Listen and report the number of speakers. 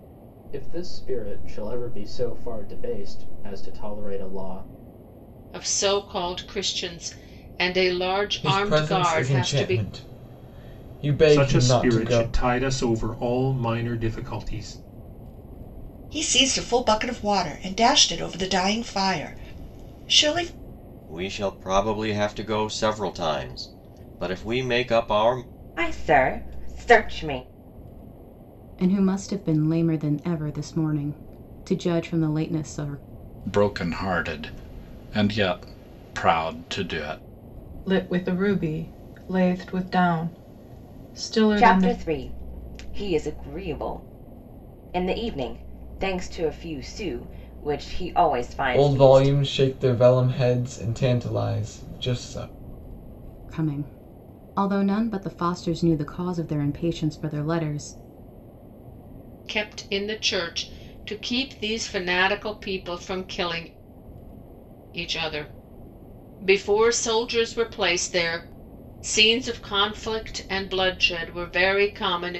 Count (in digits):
10